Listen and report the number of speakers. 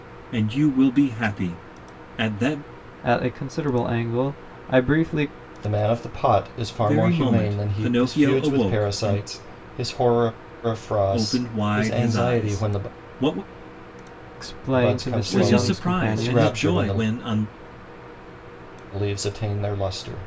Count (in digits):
3